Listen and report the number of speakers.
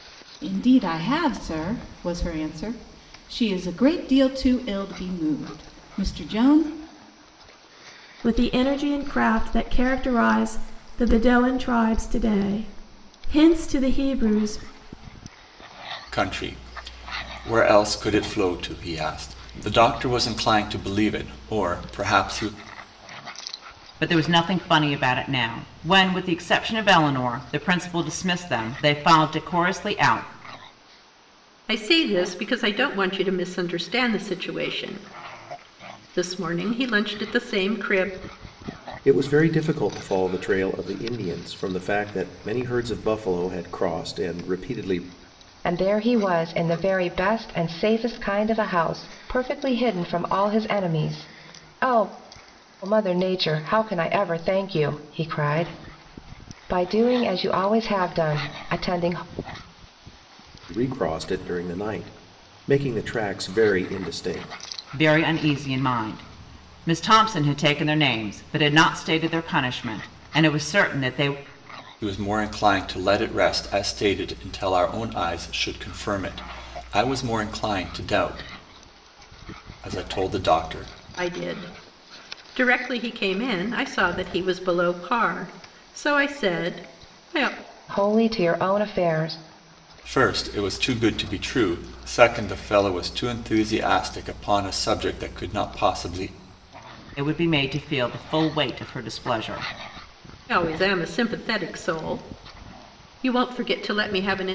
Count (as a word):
seven